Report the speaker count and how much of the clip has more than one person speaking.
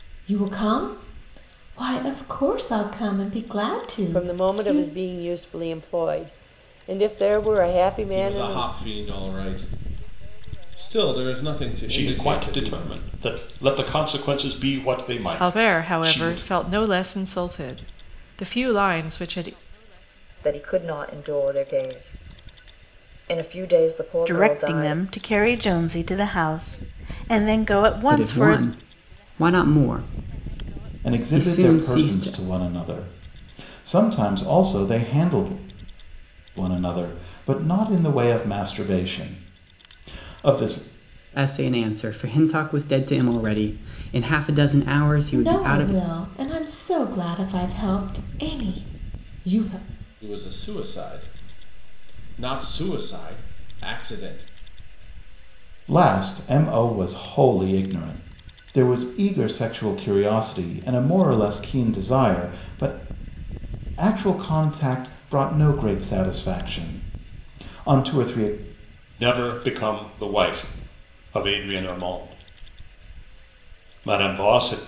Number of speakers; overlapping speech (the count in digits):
9, about 9%